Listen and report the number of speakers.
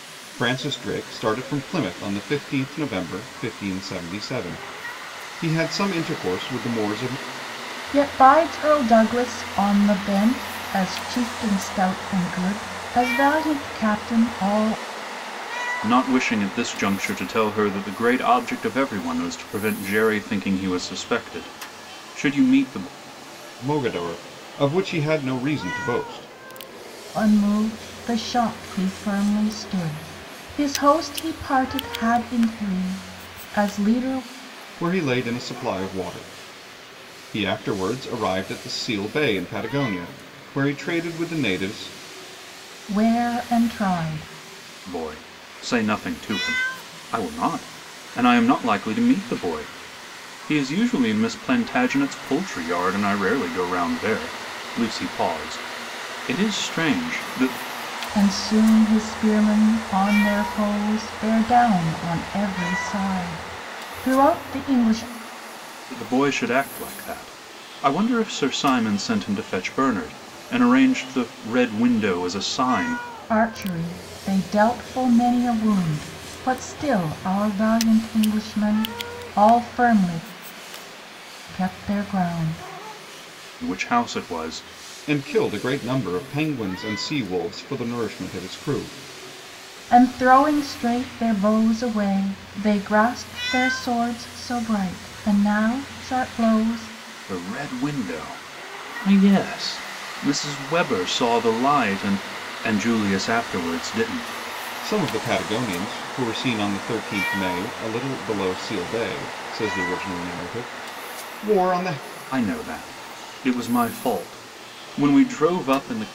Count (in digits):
3